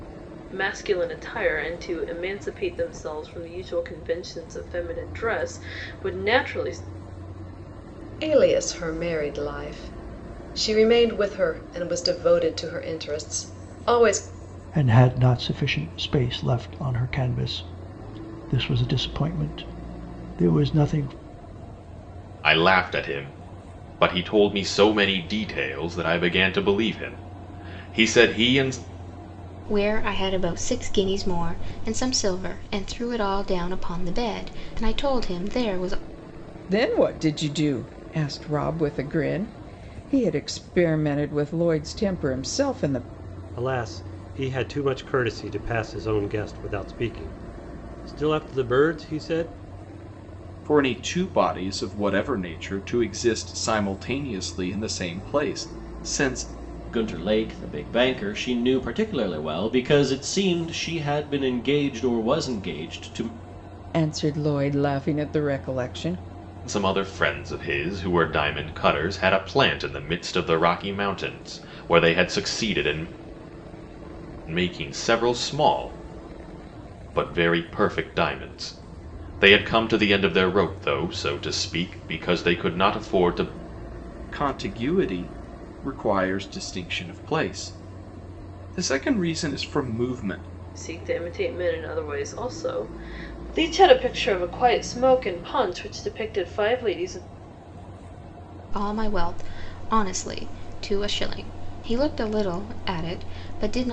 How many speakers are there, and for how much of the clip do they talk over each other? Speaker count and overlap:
nine, no overlap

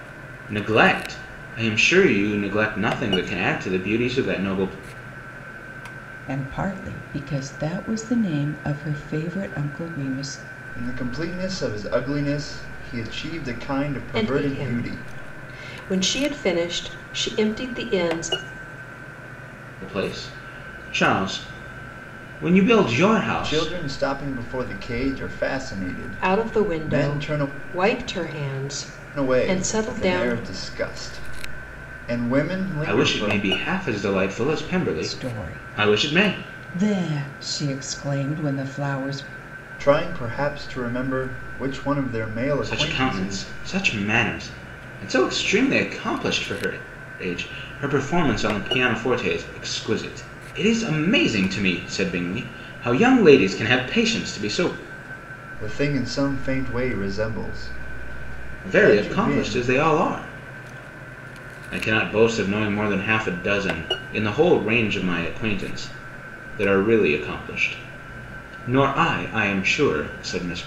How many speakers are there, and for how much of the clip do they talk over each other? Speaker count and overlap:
four, about 11%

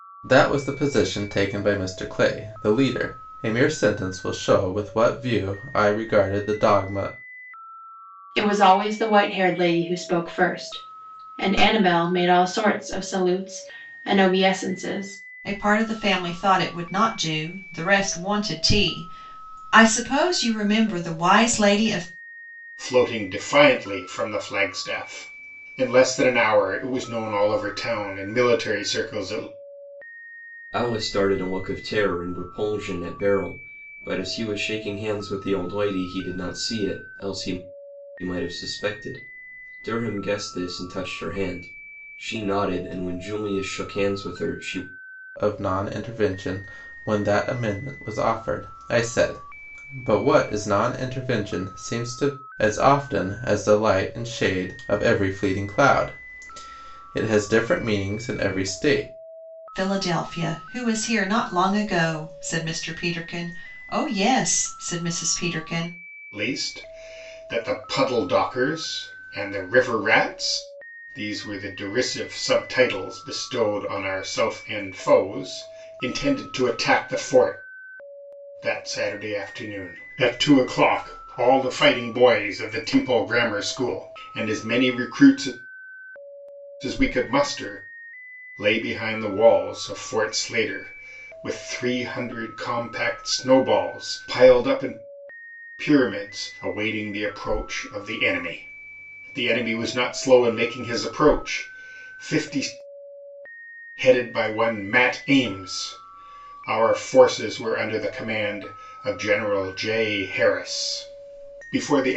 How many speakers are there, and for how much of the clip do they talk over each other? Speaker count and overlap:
five, no overlap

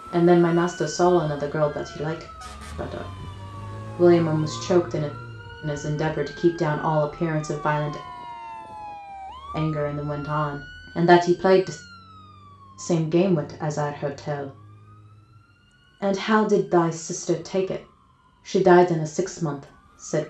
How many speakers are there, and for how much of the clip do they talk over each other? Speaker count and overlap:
one, no overlap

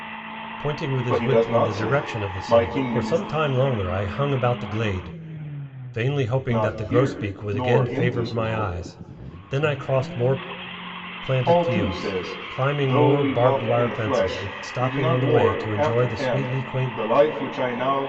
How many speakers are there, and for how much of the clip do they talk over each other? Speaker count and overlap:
two, about 55%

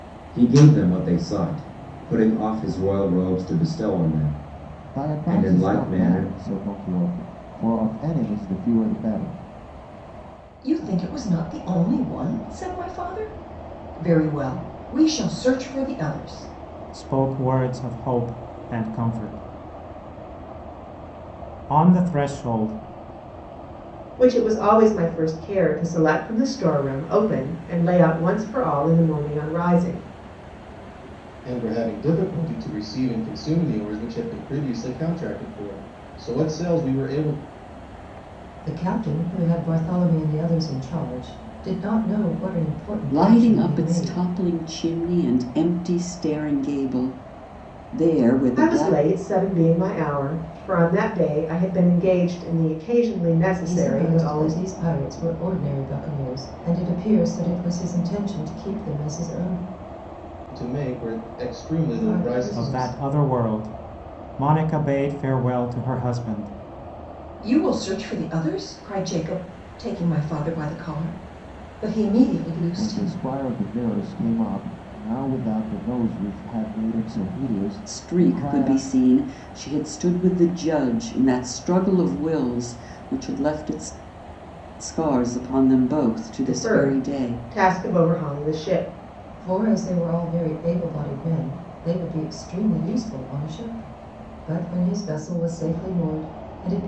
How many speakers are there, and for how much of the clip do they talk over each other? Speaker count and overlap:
eight, about 8%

